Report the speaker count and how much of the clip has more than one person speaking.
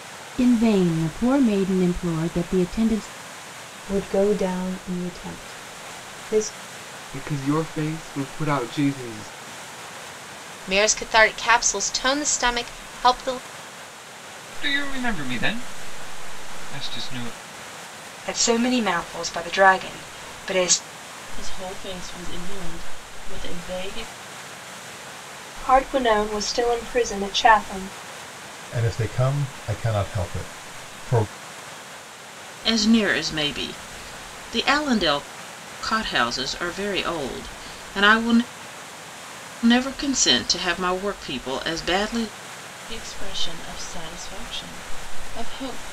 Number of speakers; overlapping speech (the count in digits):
10, no overlap